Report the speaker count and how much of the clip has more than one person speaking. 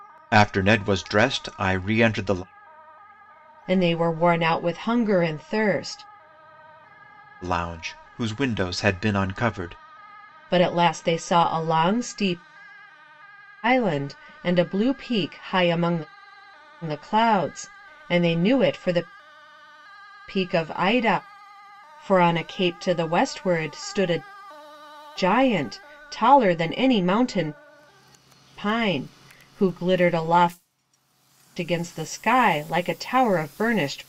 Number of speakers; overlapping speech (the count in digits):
2, no overlap